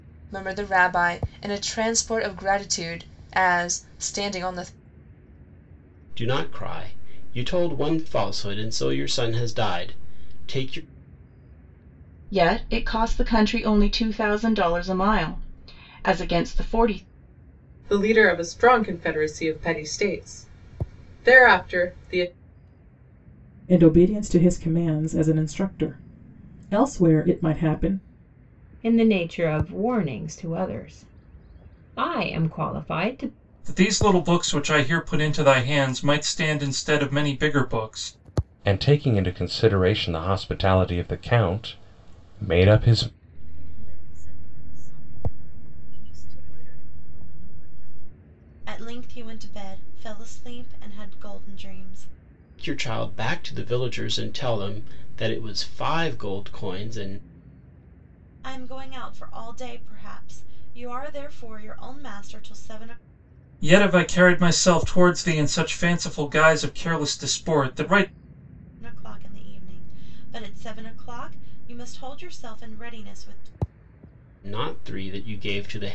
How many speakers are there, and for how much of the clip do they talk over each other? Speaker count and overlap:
ten, no overlap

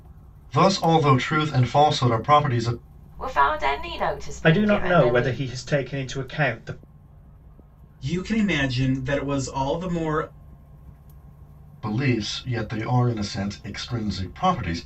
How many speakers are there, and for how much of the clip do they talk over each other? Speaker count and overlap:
four, about 6%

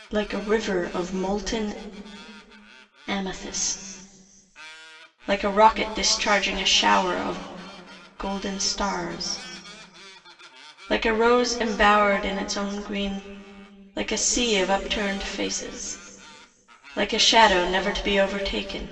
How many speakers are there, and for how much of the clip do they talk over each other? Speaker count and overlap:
one, no overlap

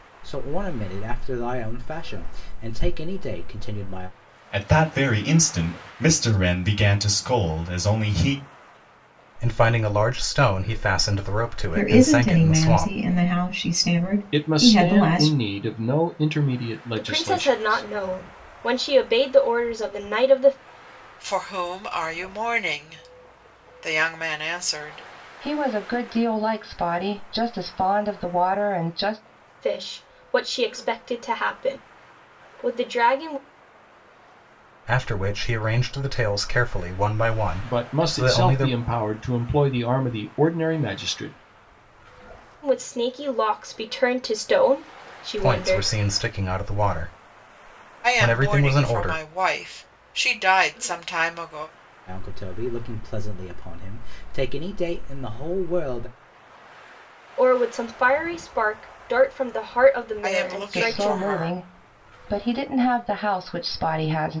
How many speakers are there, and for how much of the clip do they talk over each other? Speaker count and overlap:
eight, about 12%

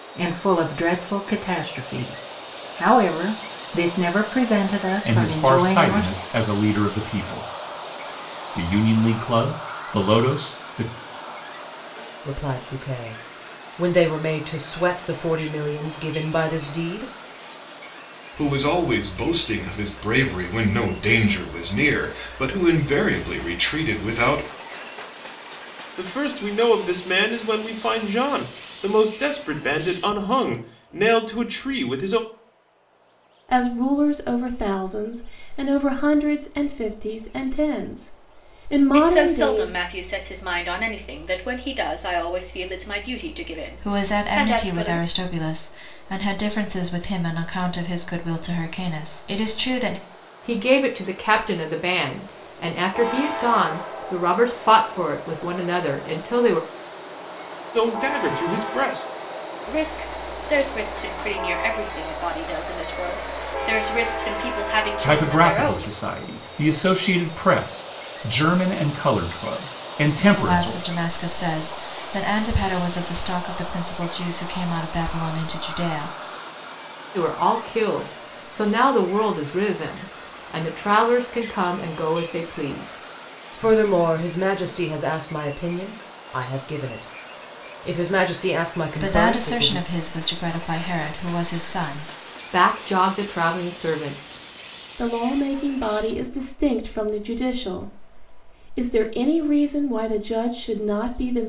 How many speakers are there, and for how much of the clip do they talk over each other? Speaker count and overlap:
nine, about 6%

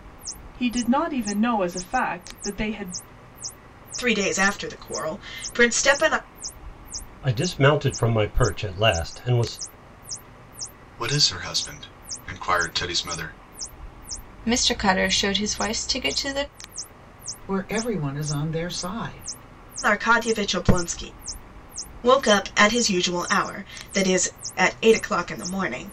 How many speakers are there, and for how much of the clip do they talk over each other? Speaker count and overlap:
six, no overlap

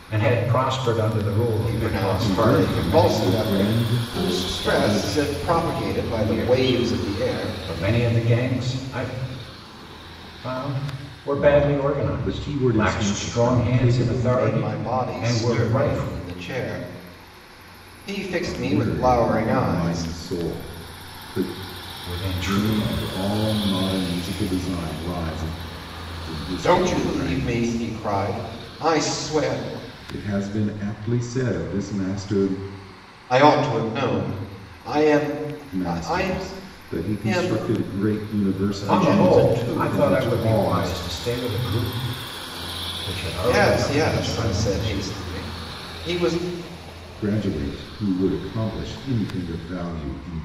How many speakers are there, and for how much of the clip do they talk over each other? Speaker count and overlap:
three, about 38%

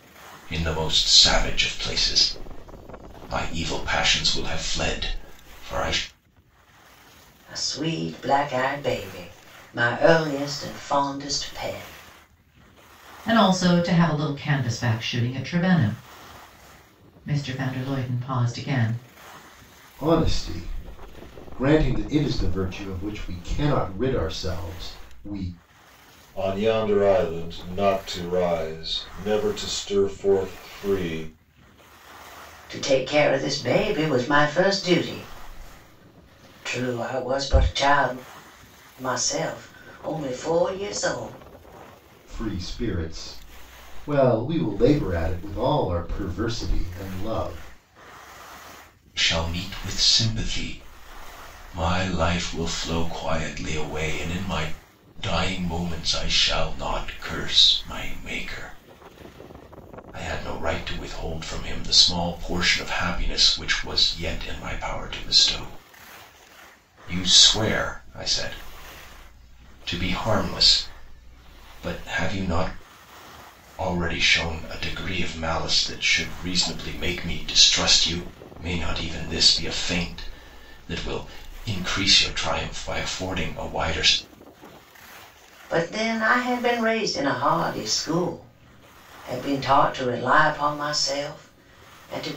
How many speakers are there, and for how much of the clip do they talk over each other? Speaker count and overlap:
five, no overlap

